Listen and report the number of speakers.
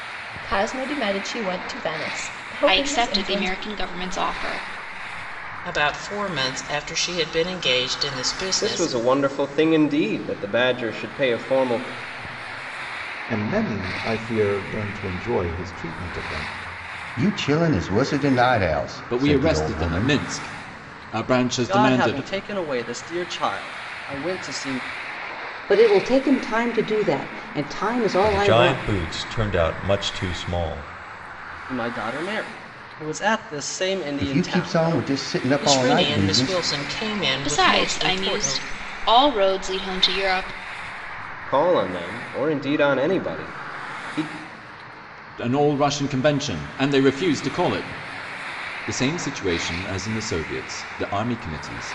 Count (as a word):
ten